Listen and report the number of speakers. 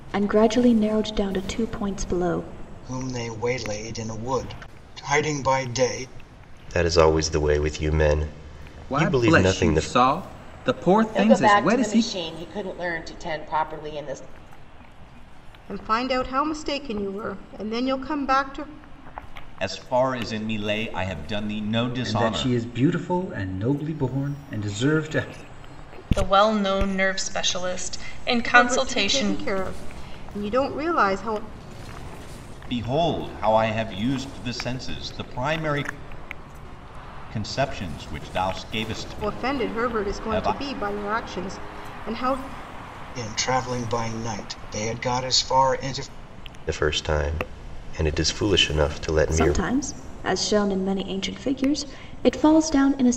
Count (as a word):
nine